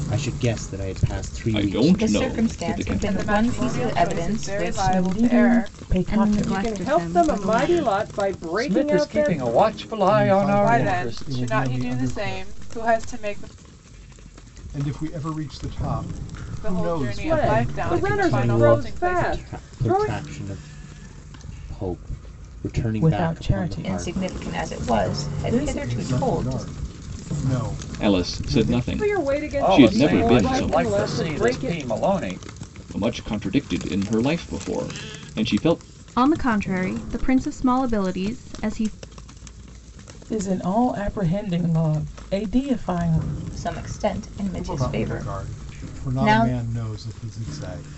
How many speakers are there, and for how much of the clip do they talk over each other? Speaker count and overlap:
9, about 47%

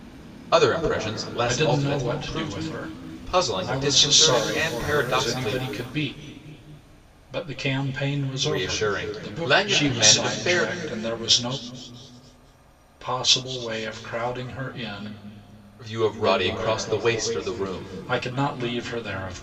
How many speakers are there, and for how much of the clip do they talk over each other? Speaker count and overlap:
2, about 36%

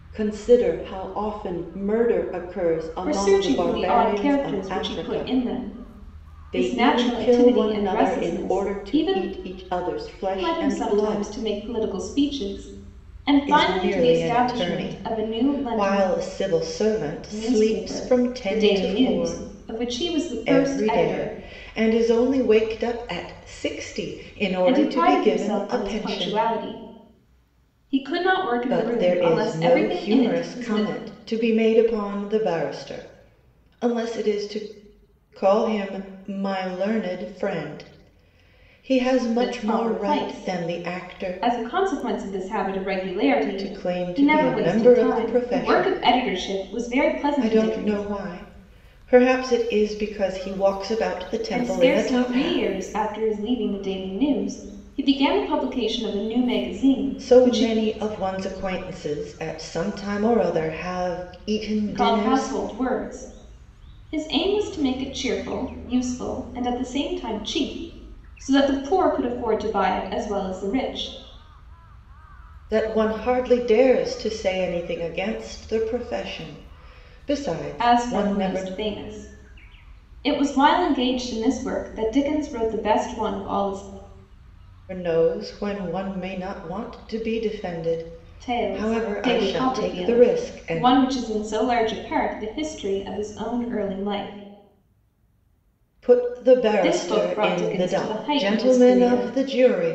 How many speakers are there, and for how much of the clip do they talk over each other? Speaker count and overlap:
2, about 29%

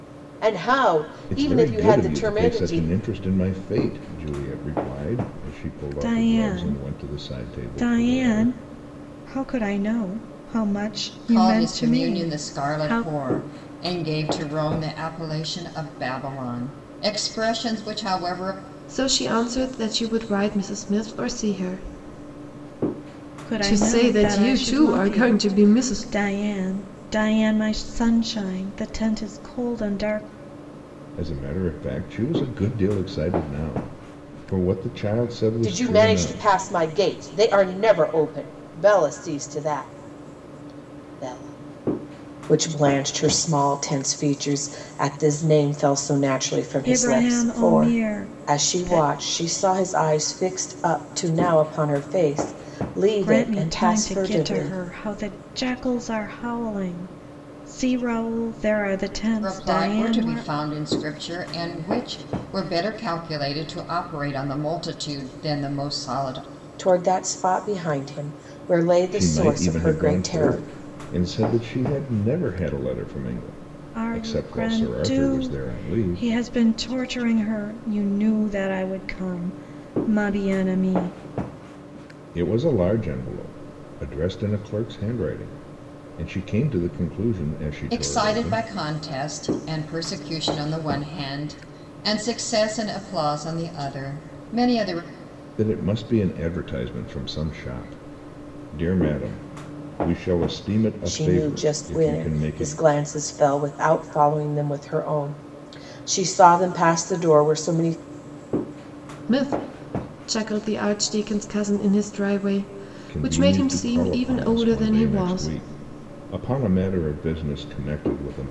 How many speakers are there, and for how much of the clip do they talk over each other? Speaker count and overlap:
5, about 20%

